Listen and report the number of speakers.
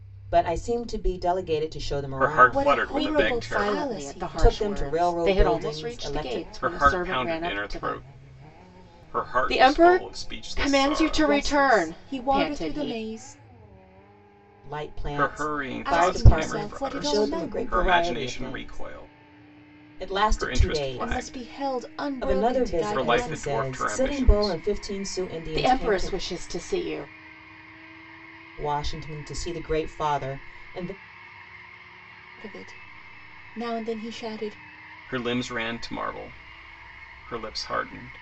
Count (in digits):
4